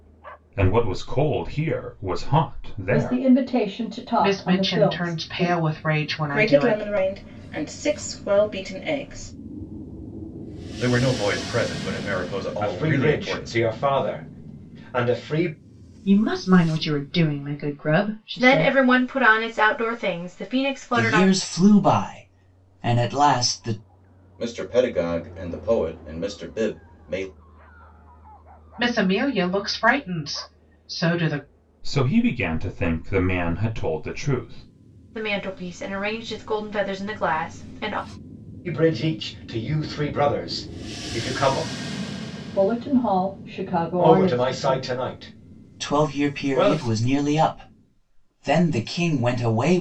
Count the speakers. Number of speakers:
10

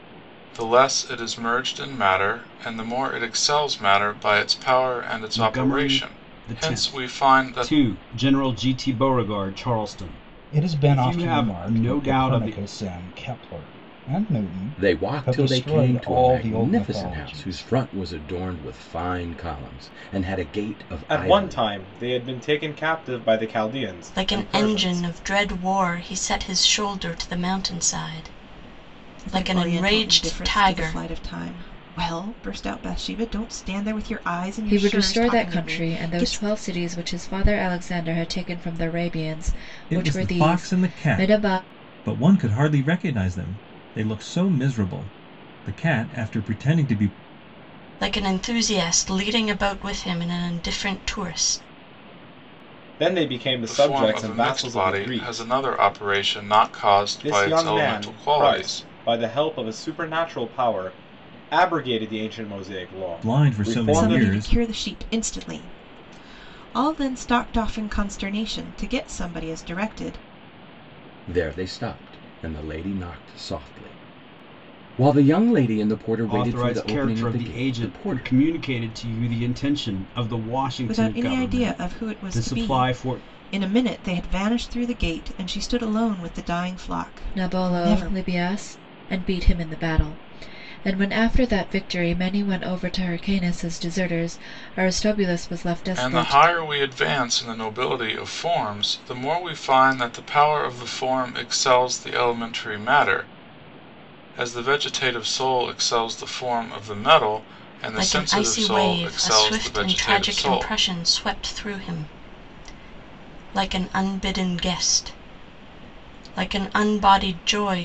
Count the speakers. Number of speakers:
9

